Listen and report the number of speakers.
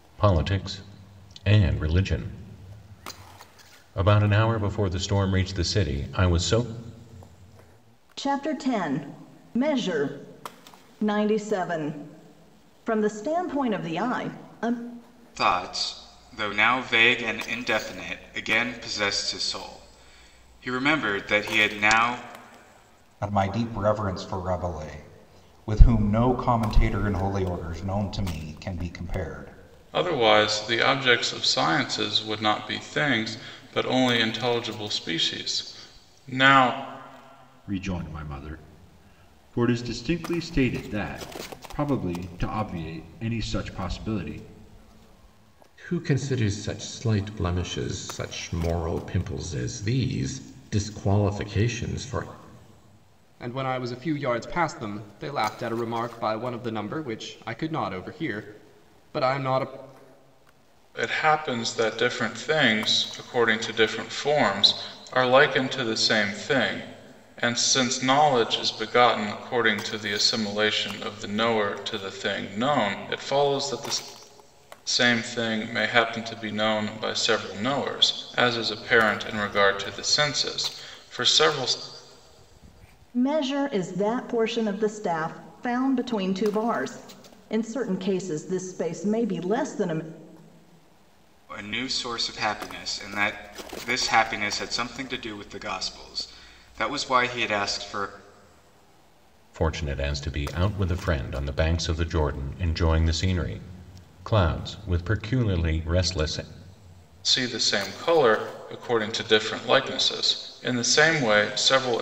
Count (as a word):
eight